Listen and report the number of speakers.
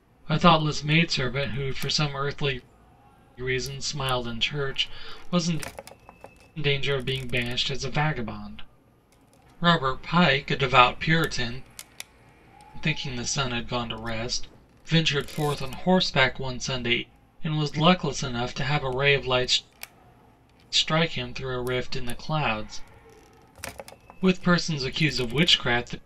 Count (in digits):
1